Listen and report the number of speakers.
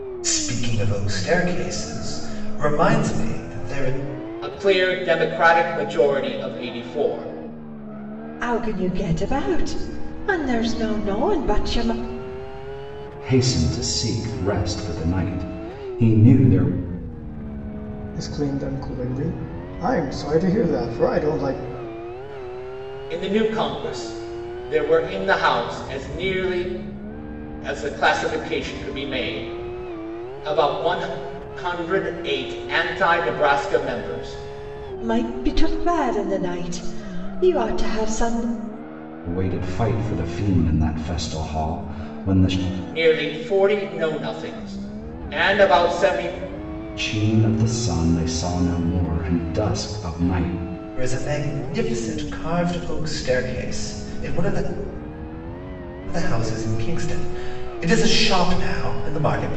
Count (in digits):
5